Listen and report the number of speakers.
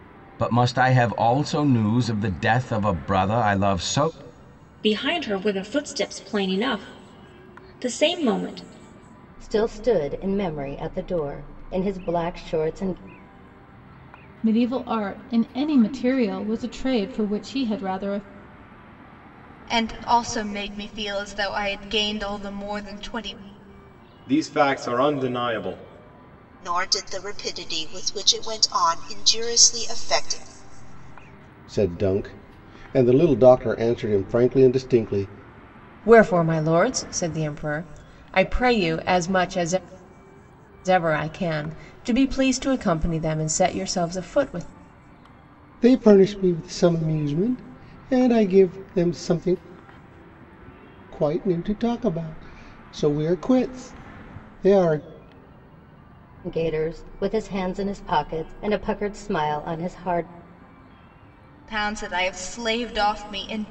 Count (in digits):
9